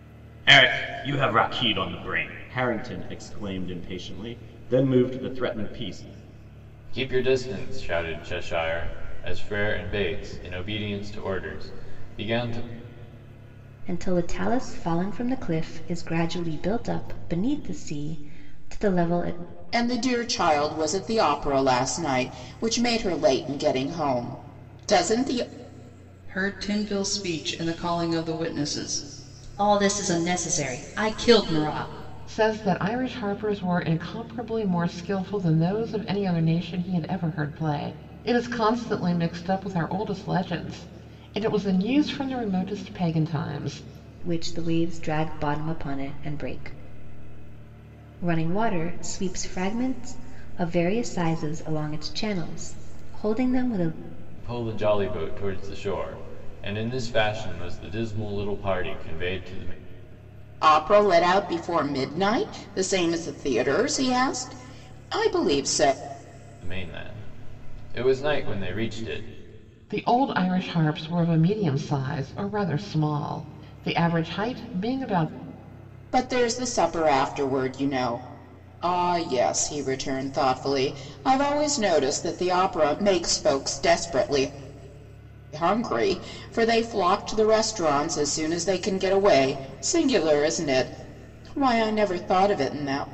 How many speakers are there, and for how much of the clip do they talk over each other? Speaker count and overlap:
six, no overlap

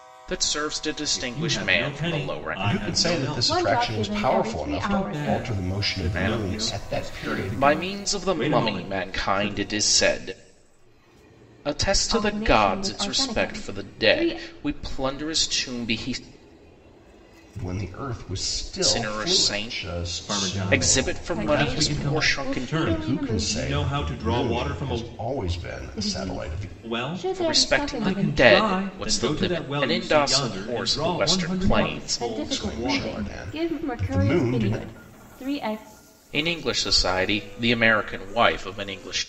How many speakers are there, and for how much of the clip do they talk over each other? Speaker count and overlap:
four, about 65%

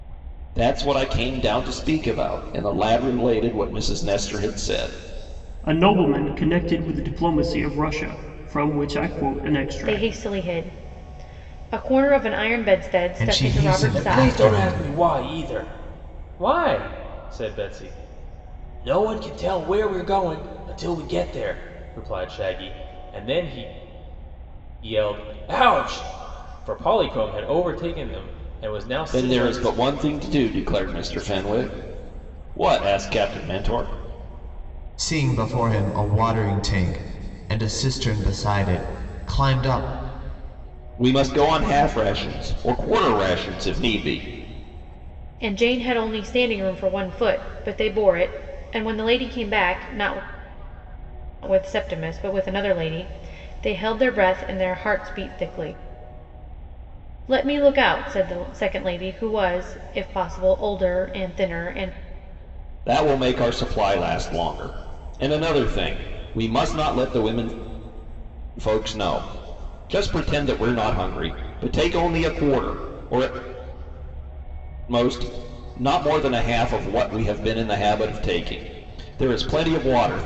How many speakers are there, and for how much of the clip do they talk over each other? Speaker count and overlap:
five, about 4%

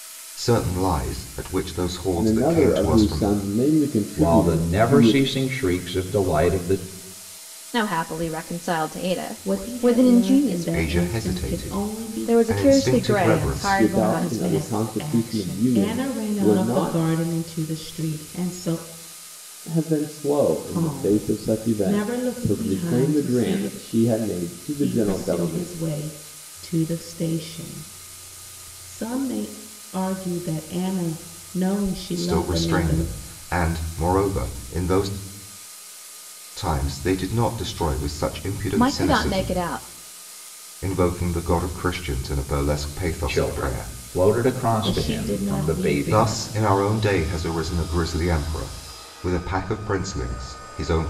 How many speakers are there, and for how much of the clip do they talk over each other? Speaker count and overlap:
five, about 36%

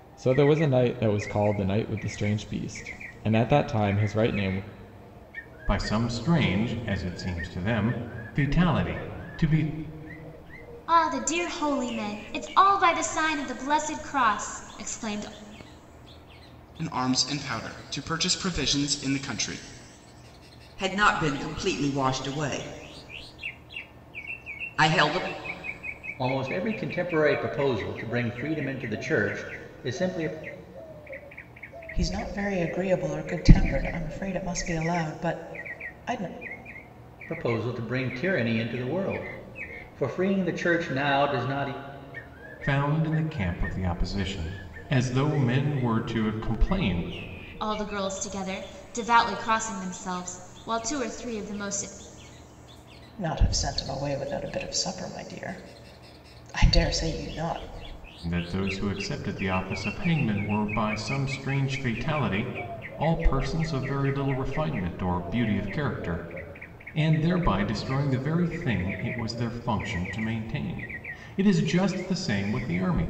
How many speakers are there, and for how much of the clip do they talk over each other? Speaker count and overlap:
seven, no overlap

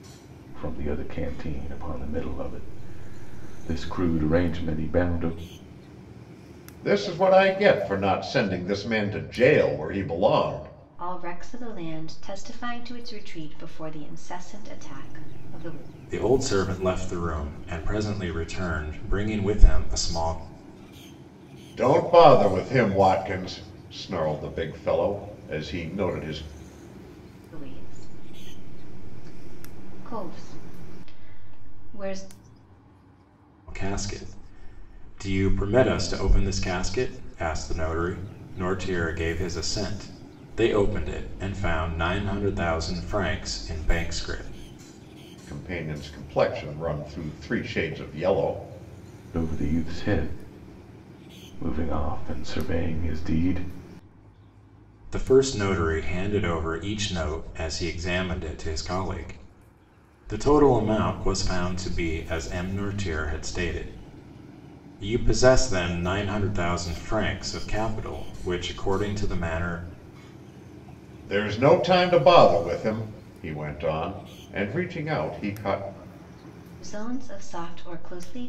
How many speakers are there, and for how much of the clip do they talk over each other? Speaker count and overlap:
four, no overlap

